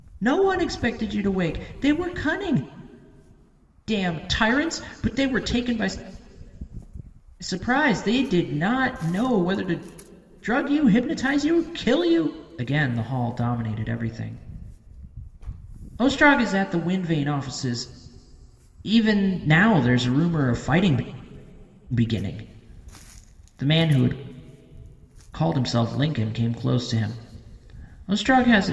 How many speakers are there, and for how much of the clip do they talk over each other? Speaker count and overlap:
1, no overlap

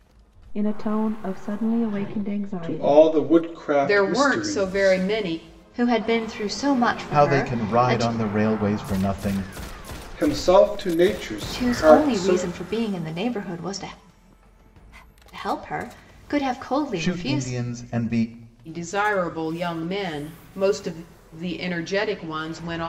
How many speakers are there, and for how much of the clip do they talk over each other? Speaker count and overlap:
5, about 19%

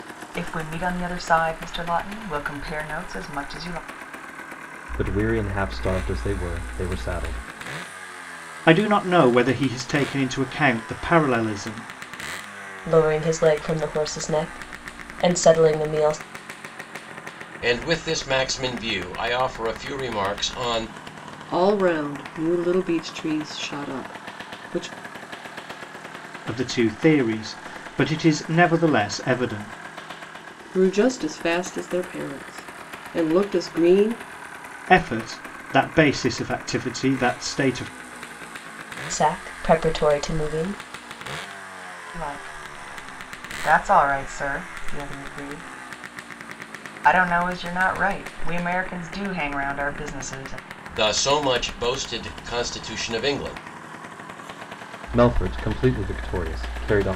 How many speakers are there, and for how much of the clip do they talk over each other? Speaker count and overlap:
6, no overlap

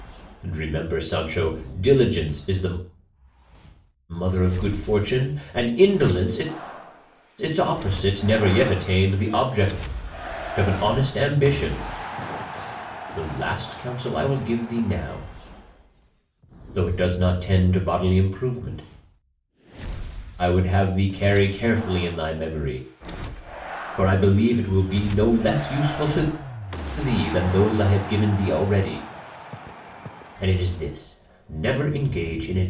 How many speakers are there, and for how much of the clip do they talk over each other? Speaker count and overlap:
1, no overlap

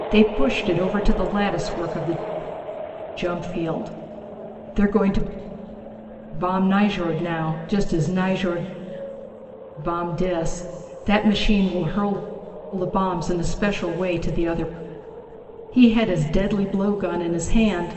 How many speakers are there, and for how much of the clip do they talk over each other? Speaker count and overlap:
1, no overlap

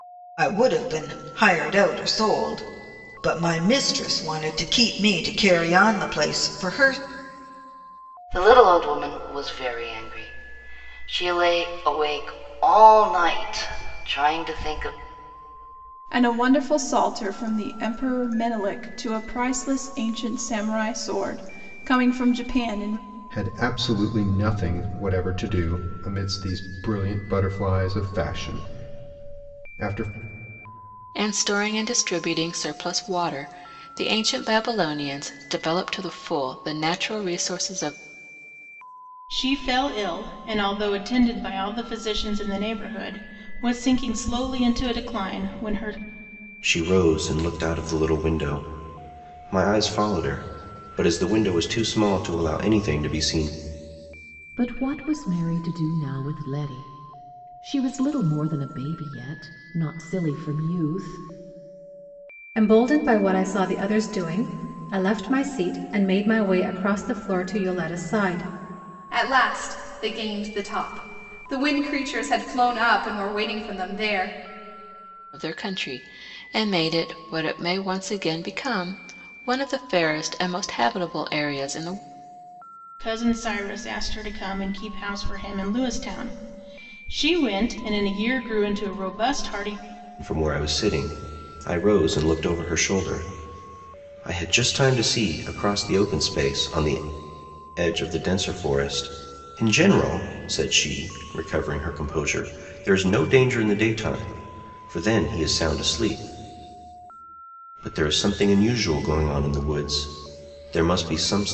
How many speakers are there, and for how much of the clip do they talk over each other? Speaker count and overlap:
10, no overlap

